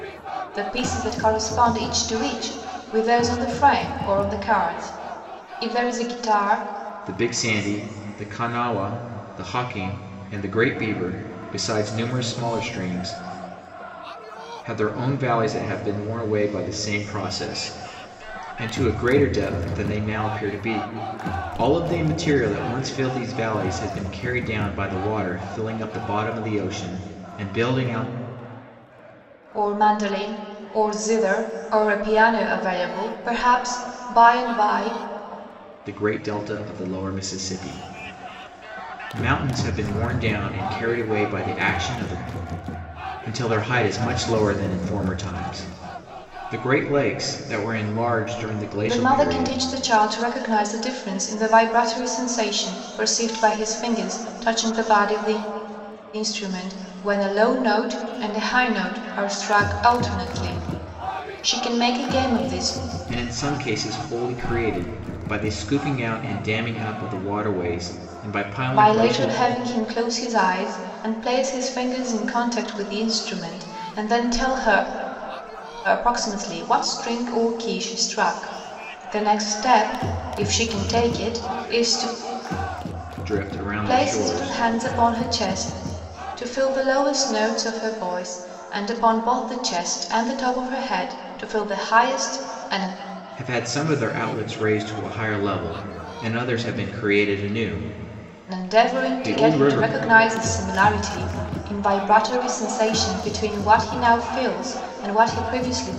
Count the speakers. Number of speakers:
2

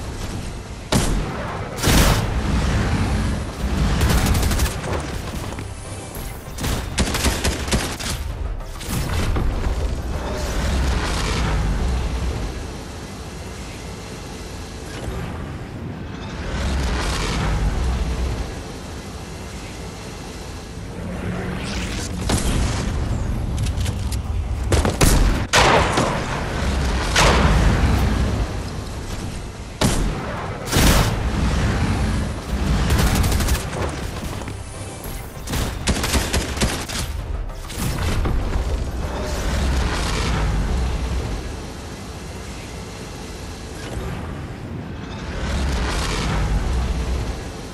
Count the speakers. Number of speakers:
0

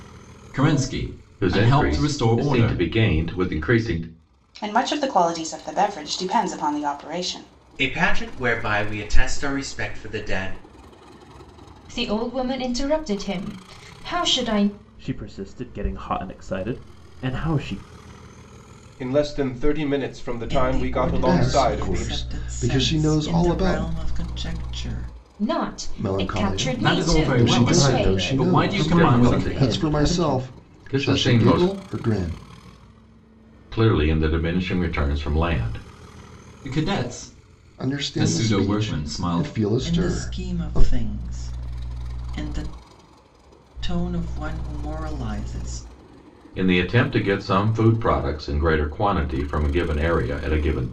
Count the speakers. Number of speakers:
9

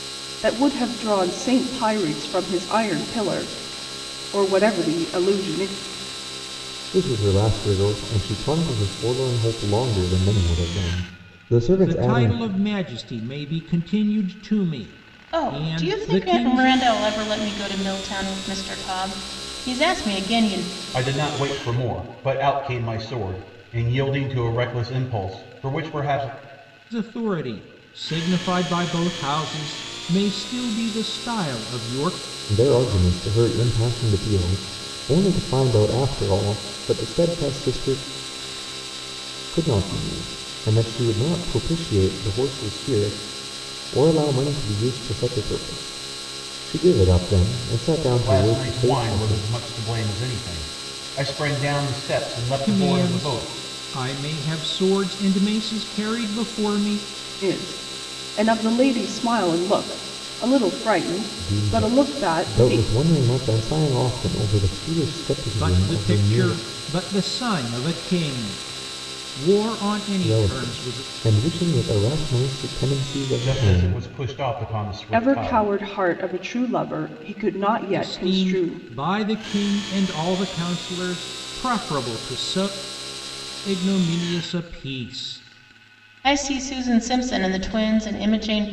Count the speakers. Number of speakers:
5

